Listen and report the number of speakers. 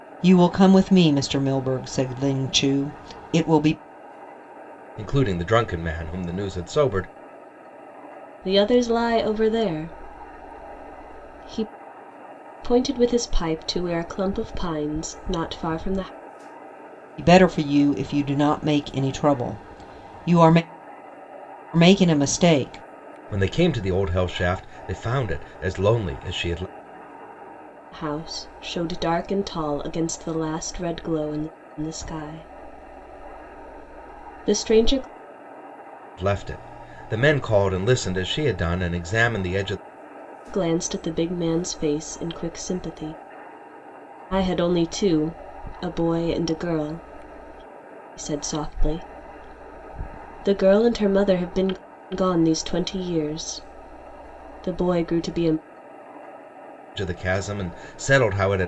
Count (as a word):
three